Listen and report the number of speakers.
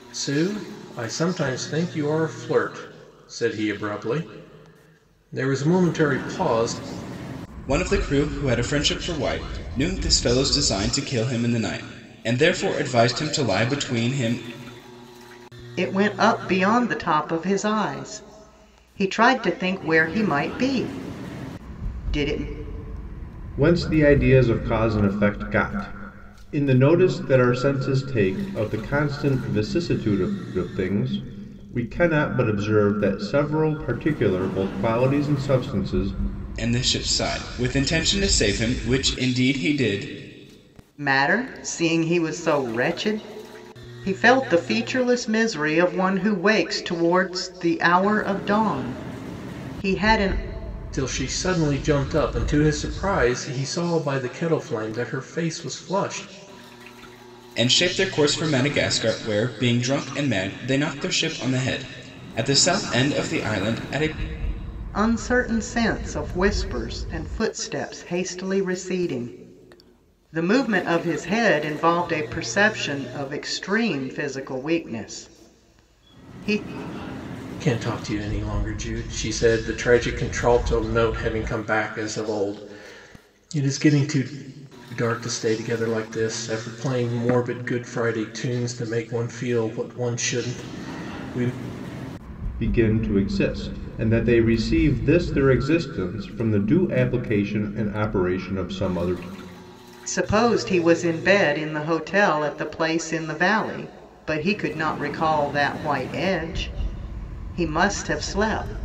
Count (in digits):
4